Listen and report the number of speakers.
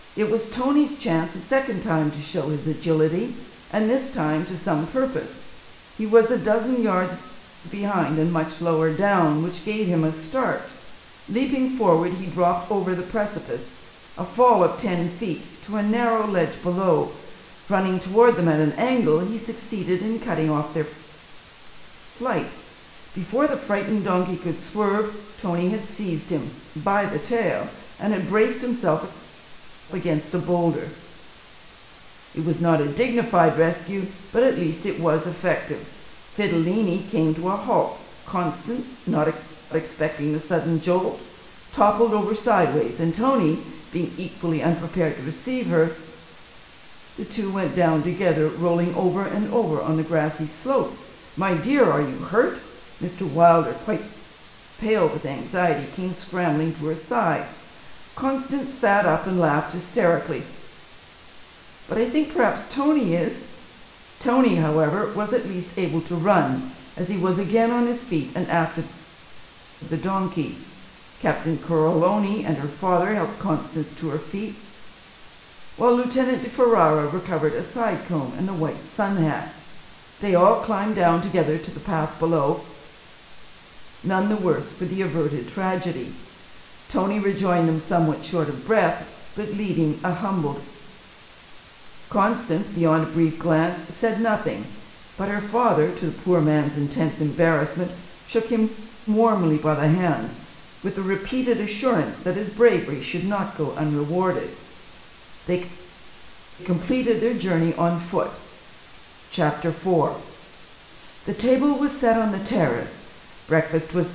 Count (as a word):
one